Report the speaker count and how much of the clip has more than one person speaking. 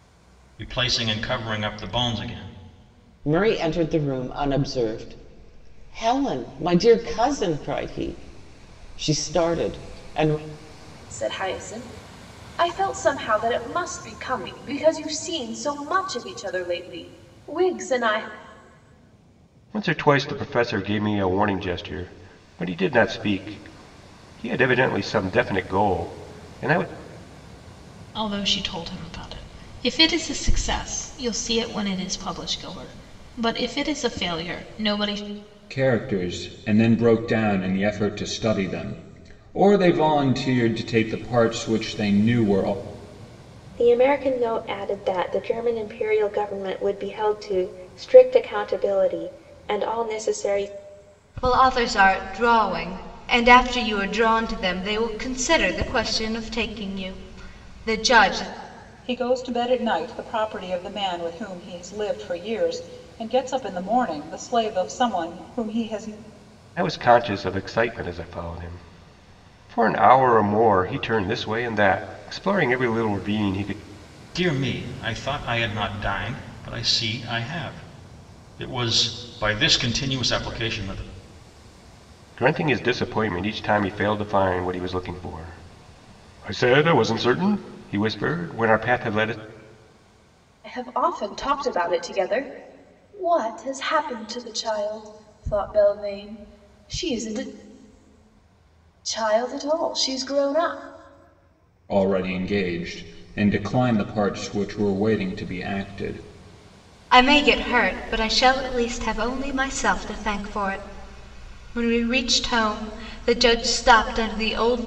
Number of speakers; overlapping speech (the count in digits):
9, no overlap